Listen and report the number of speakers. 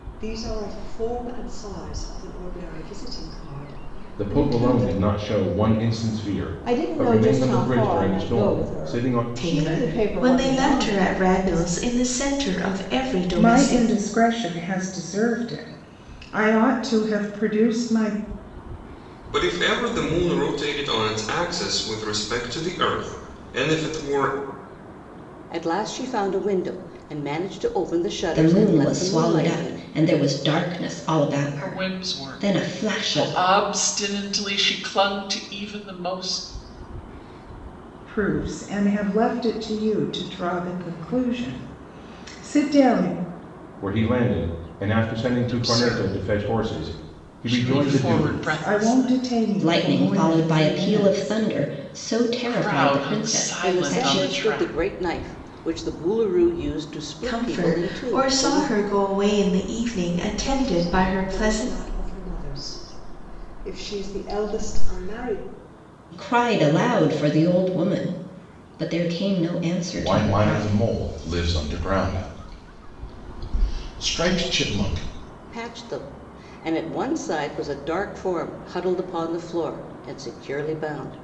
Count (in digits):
9